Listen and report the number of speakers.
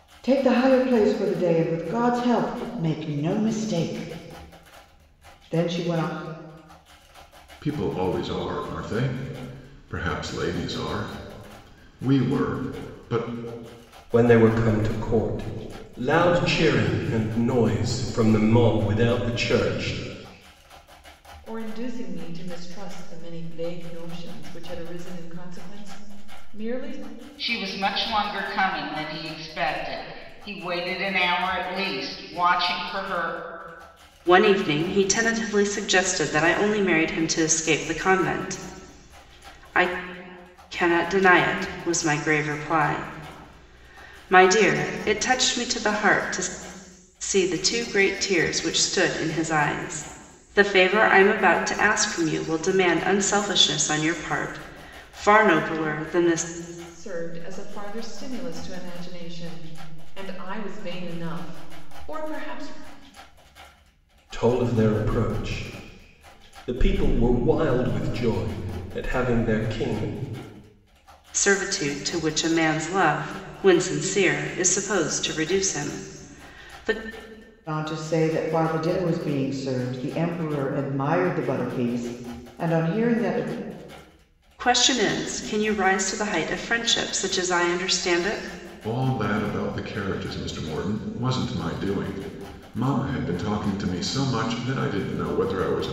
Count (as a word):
six